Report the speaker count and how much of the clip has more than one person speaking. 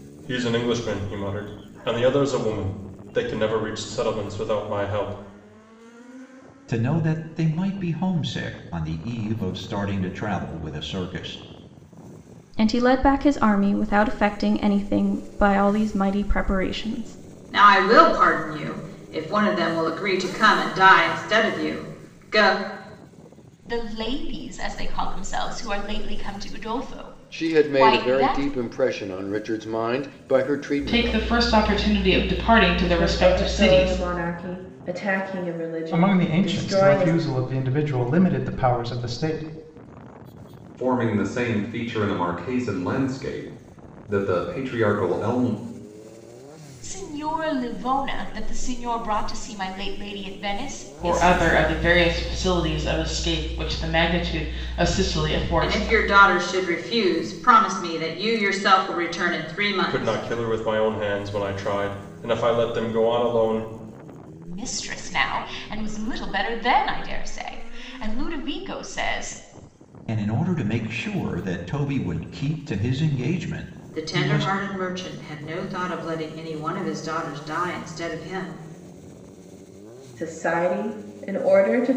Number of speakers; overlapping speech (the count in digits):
10, about 9%